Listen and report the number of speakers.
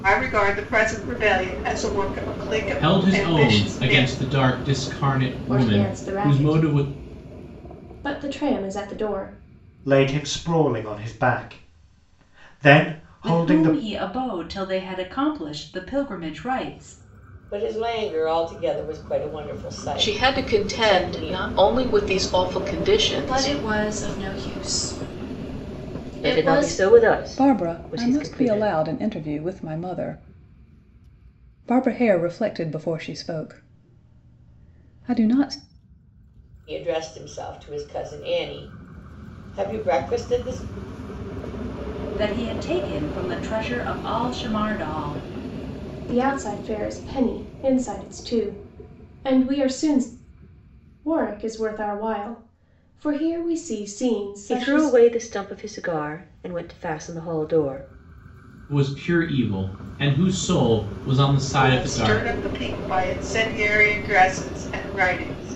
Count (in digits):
10